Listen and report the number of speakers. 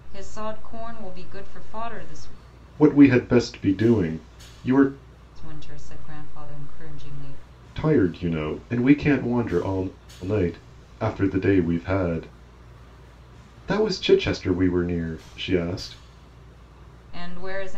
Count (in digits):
2